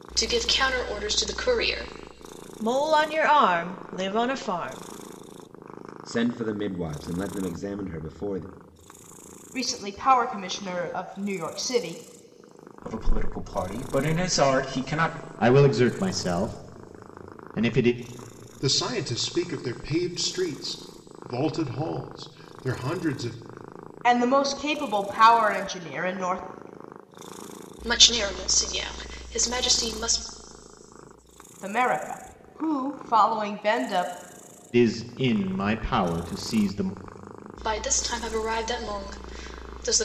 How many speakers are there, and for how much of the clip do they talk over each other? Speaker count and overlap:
seven, no overlap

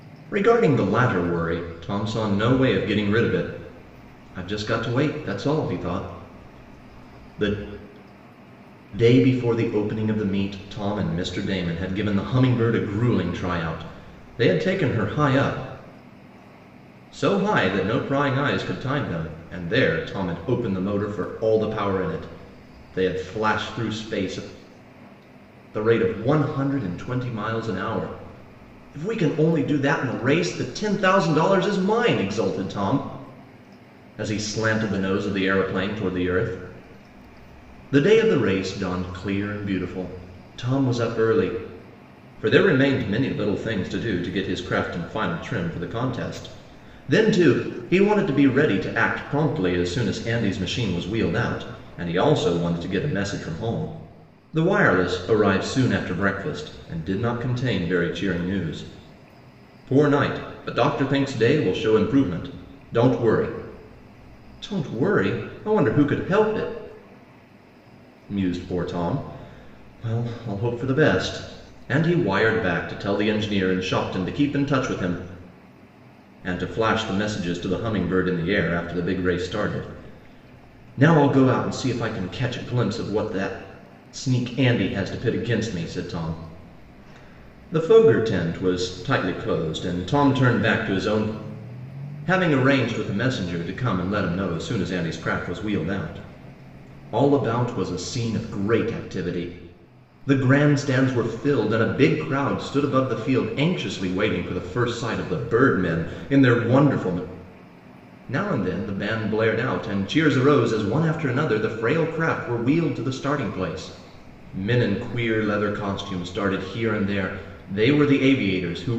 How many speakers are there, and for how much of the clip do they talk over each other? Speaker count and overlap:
one, no overlap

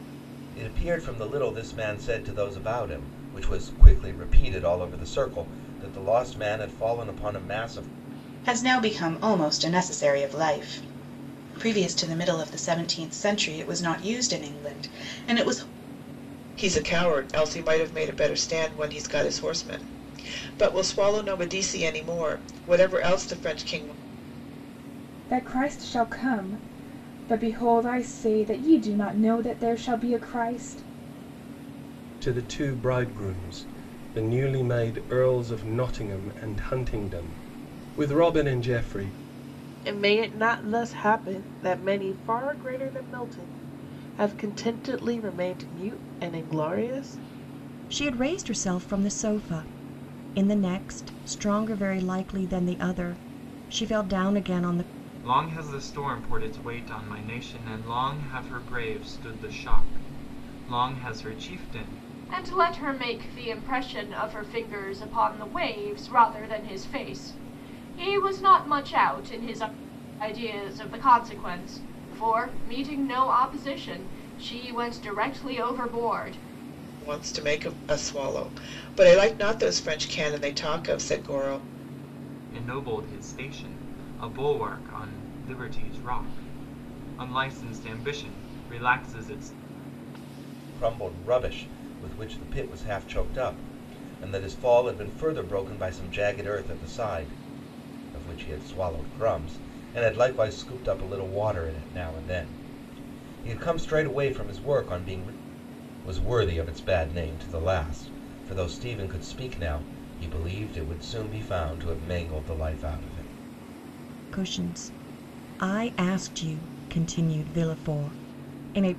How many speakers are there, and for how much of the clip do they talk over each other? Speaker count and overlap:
nine, no overlap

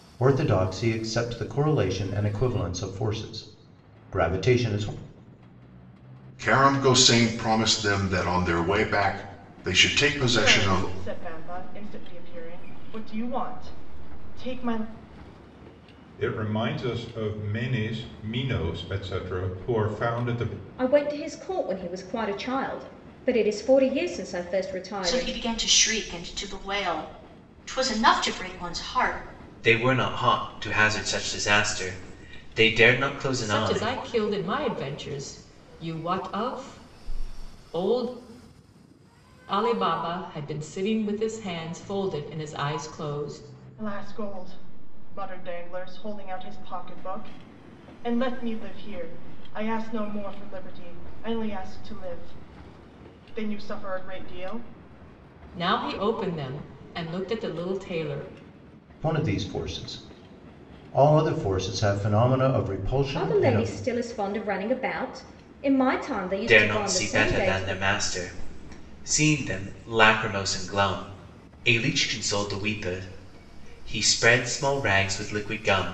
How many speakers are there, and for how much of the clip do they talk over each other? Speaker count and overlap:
eight, about 5%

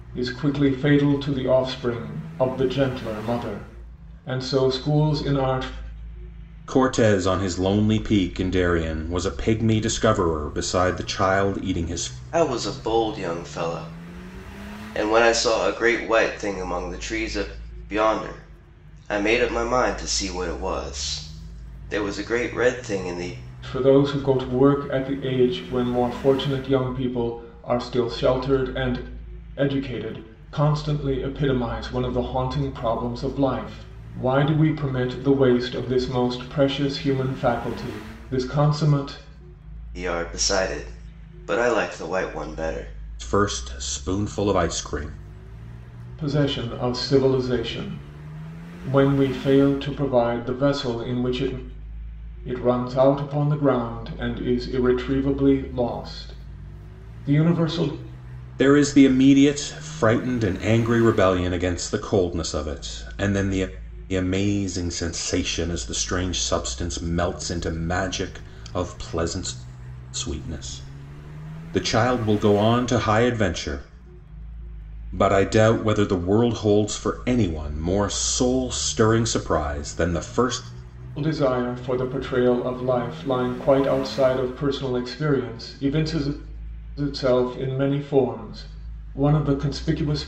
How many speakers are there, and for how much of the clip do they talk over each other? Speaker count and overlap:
three, no overlap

